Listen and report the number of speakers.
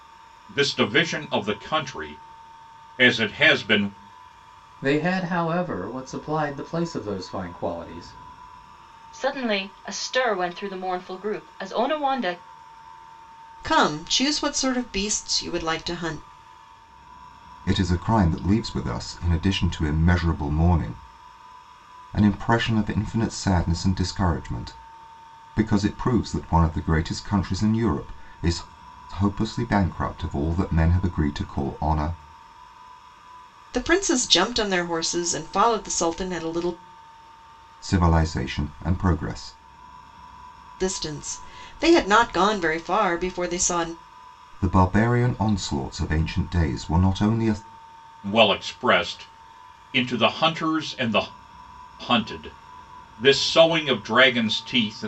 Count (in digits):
5